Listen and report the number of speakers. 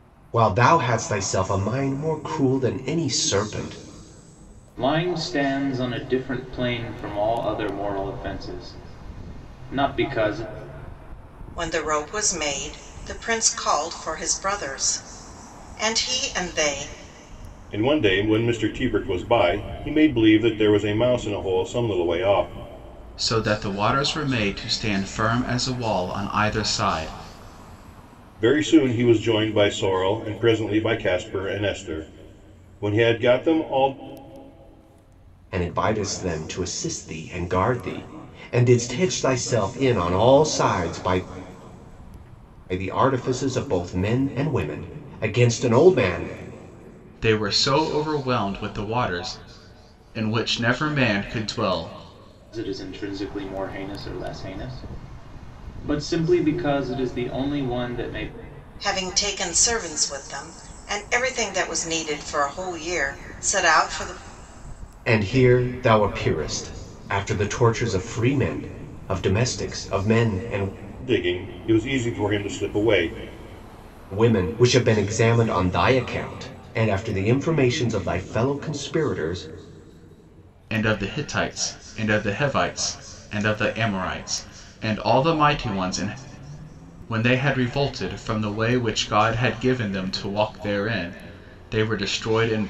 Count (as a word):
five